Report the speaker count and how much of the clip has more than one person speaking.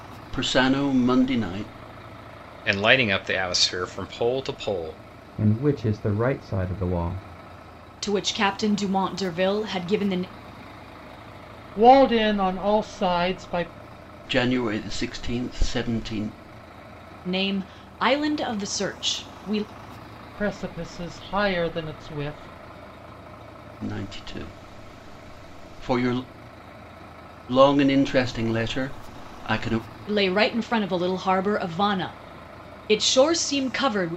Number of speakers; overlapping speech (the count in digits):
5, no overlap